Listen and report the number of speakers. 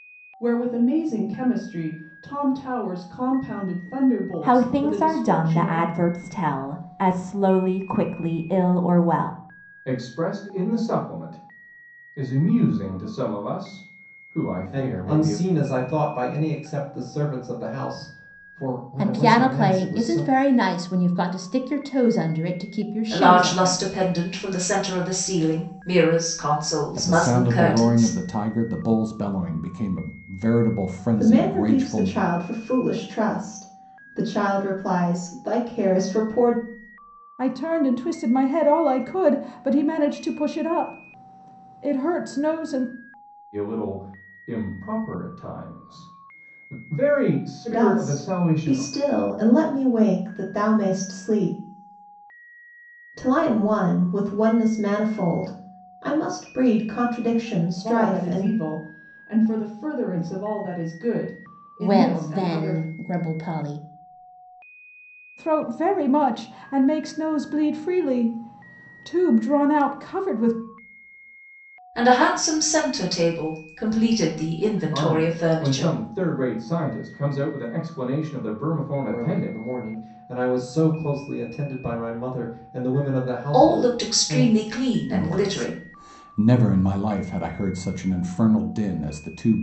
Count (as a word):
nine